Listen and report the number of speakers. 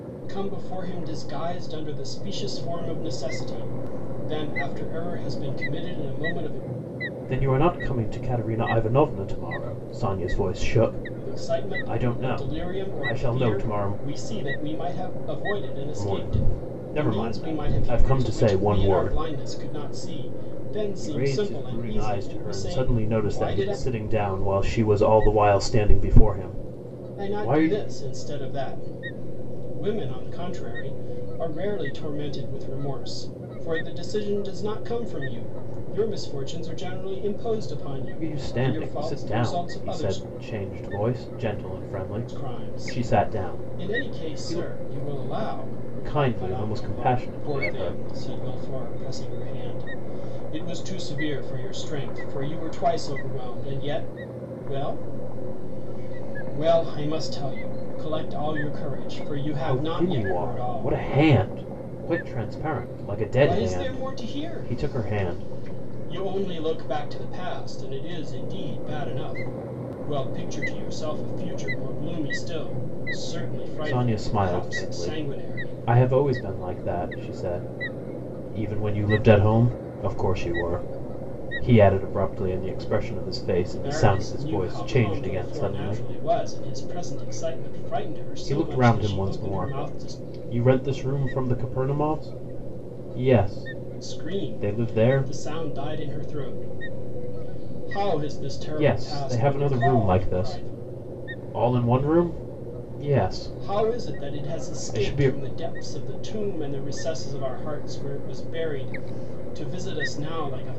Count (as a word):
two